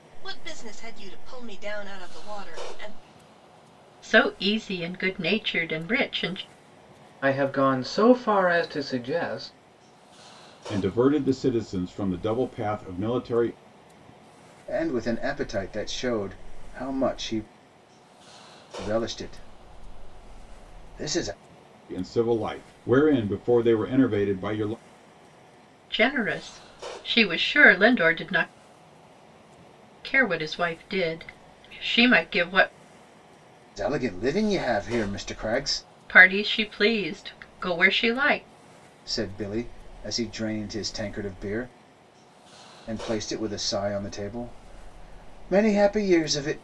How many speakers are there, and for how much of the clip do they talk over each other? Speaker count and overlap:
5, no overlap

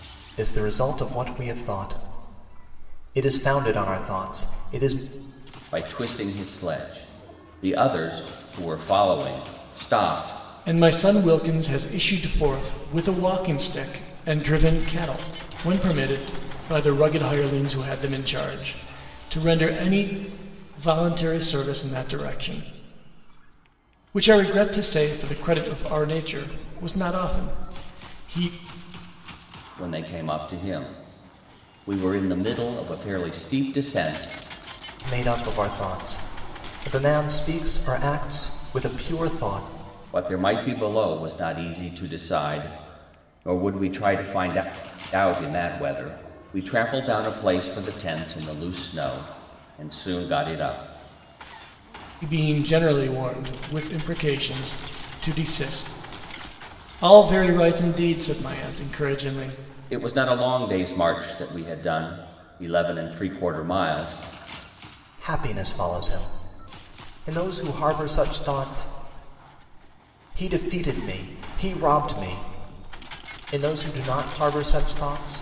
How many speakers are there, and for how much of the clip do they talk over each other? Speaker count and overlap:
3, no overlap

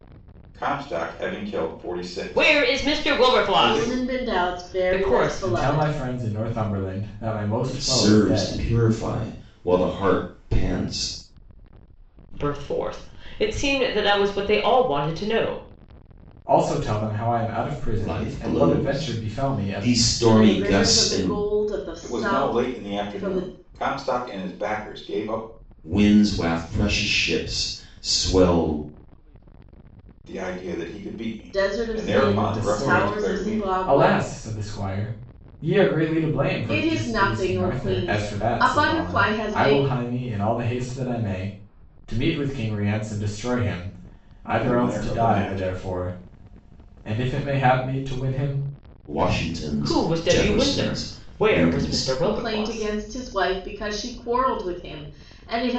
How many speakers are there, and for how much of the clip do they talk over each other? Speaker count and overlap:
5, about 34%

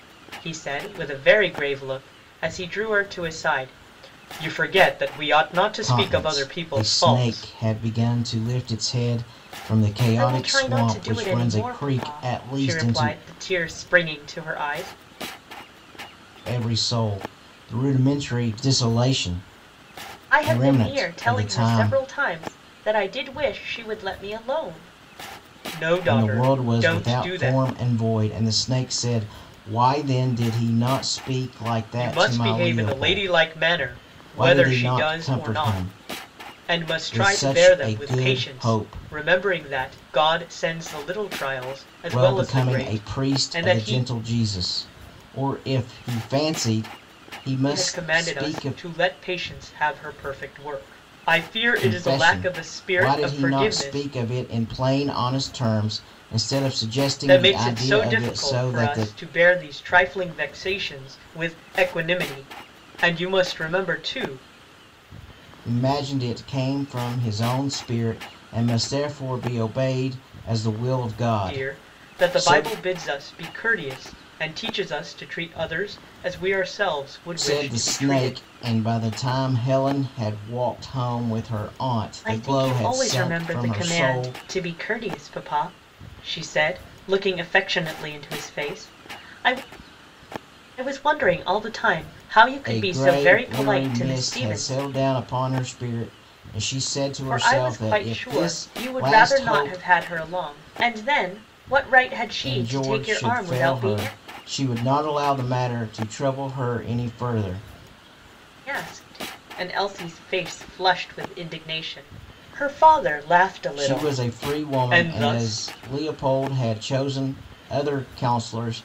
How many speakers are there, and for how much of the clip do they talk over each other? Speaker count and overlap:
2, about 29%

